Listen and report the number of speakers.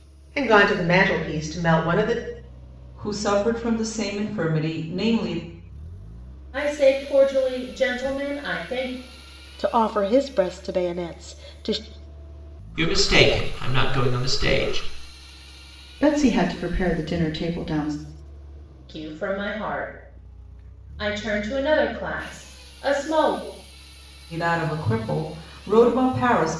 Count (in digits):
6